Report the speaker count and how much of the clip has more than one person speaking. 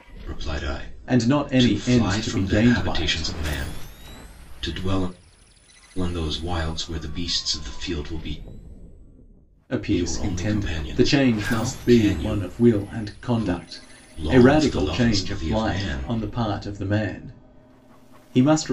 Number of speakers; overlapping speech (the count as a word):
two, about 41%